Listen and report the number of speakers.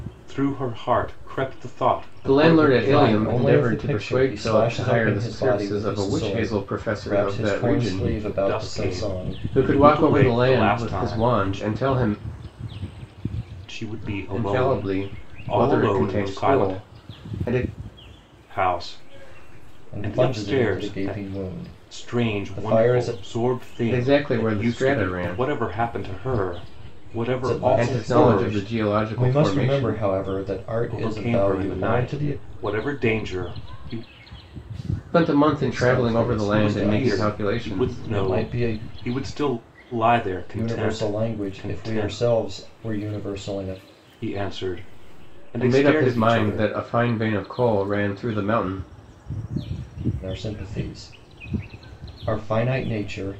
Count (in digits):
3